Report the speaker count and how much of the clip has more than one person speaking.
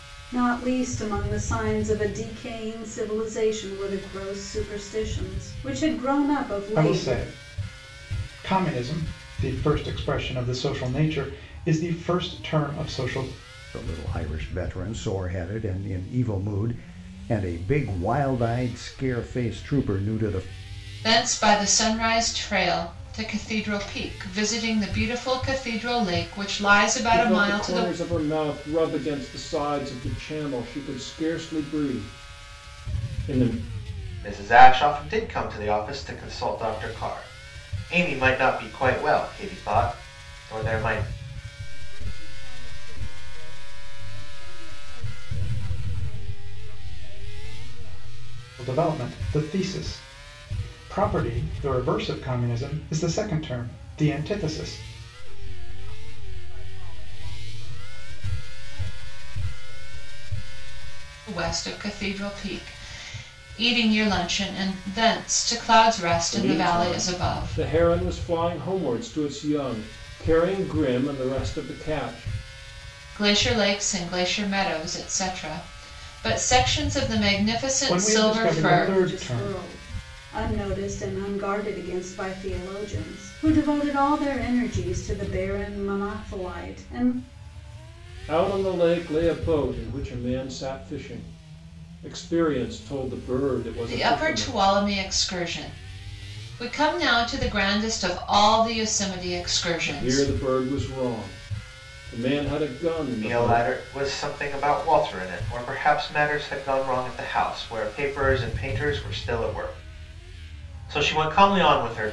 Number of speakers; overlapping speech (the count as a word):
seven, about 6%